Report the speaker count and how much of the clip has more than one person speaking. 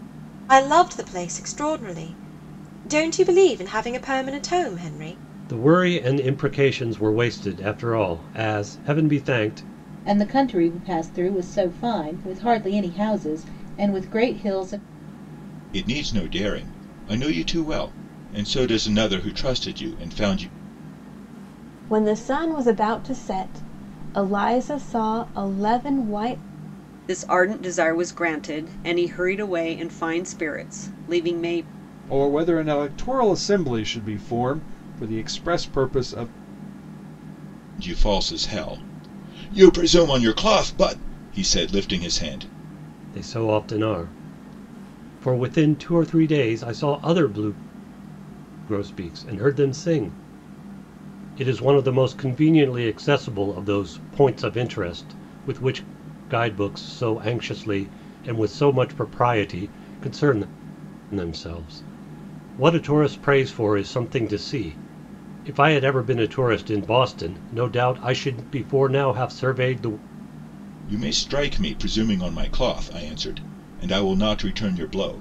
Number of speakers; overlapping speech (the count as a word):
seven, no overlap